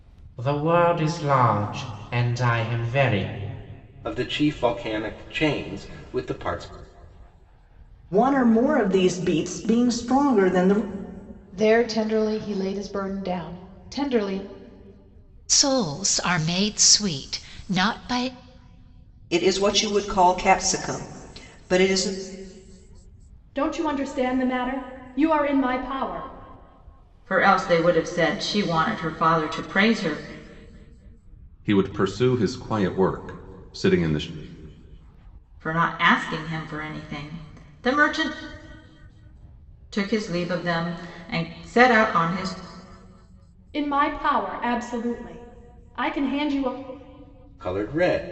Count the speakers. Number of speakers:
nine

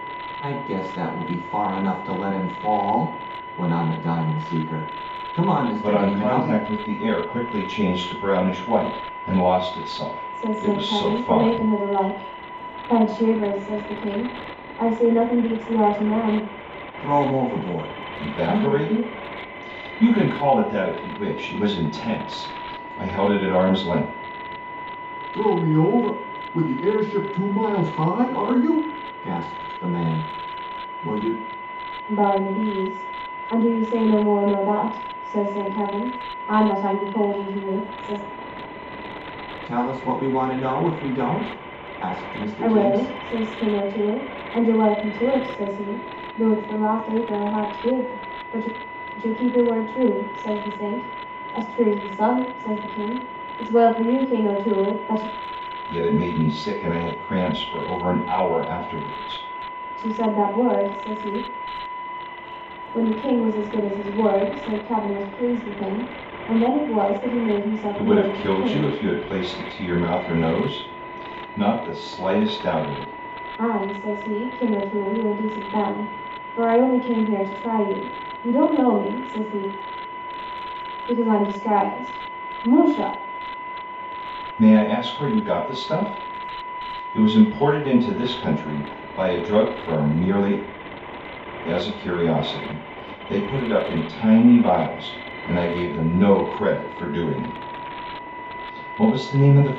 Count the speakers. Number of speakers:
three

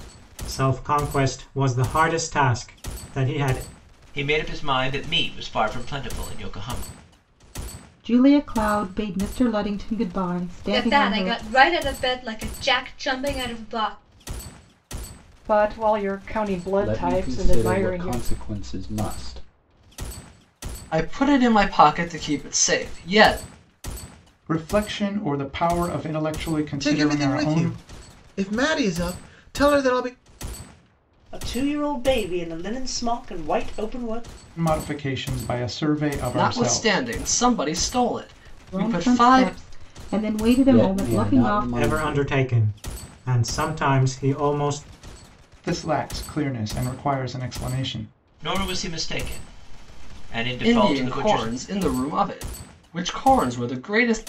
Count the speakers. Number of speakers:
ten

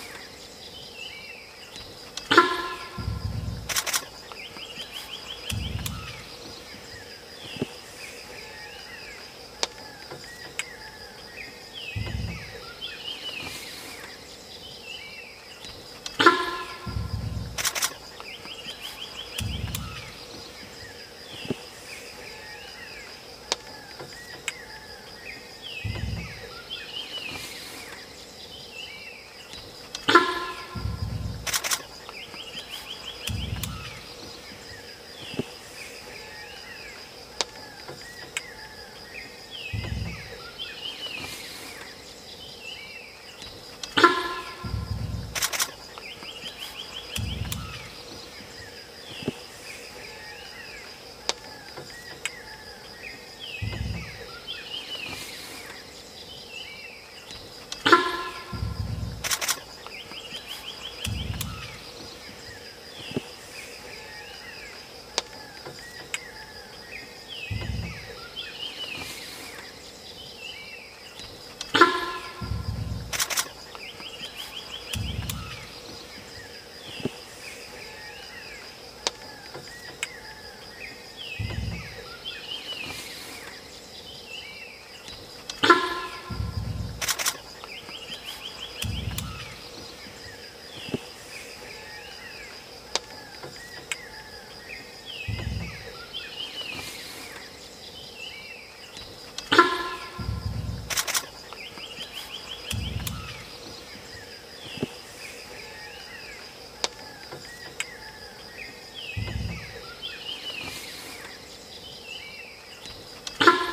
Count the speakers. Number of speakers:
zero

